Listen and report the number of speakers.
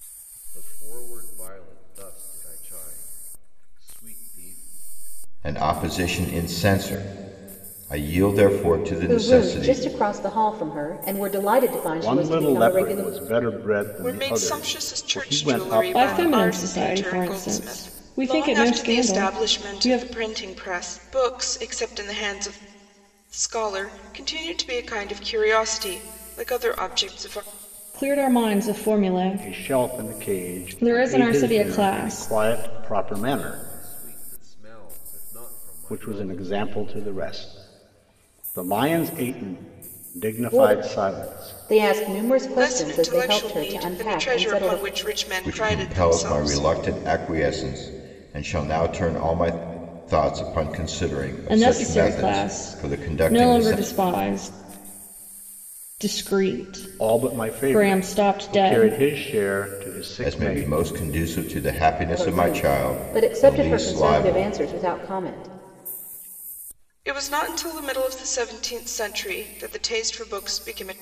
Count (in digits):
6